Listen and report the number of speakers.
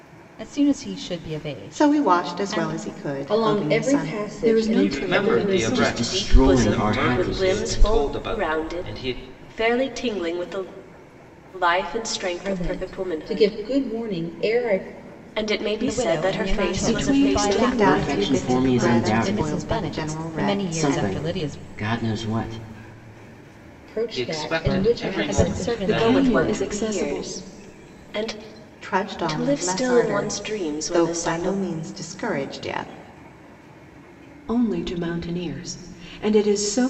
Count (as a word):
seven